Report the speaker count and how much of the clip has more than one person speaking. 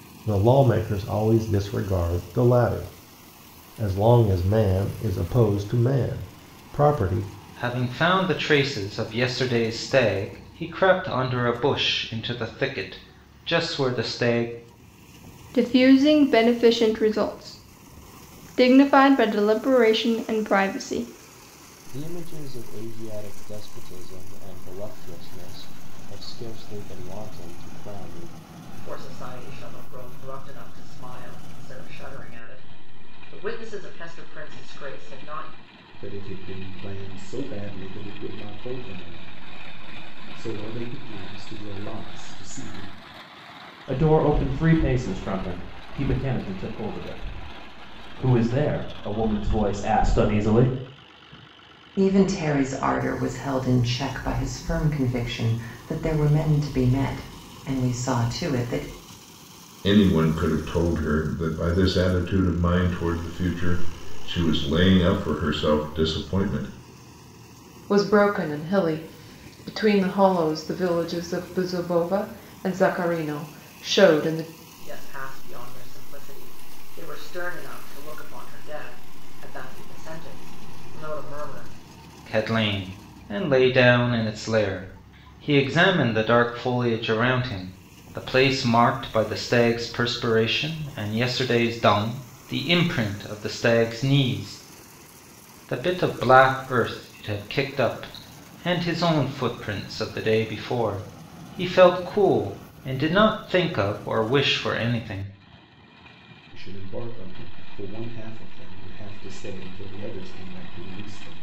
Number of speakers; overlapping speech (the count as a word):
ten, no overlap